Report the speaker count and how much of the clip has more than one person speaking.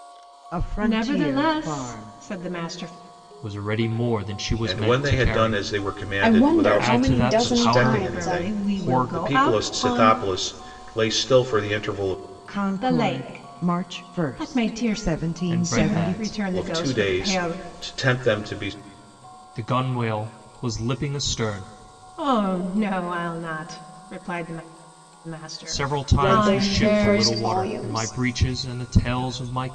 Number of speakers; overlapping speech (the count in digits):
5, about 44%